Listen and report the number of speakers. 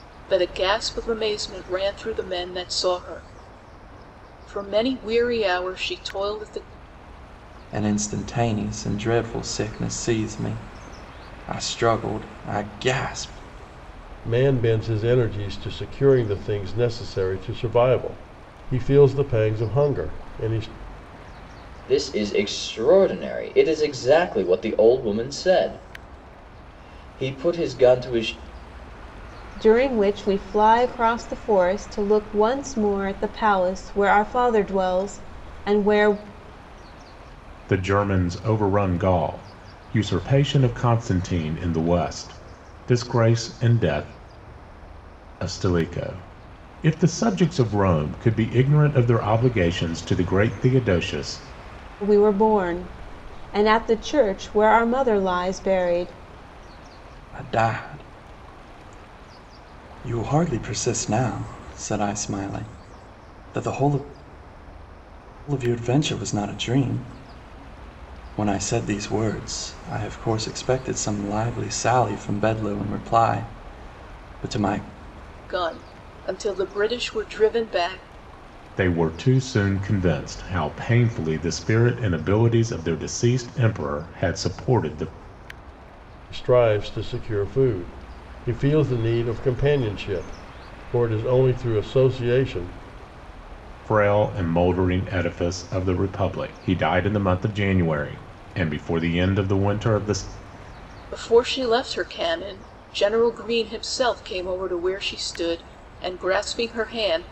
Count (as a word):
six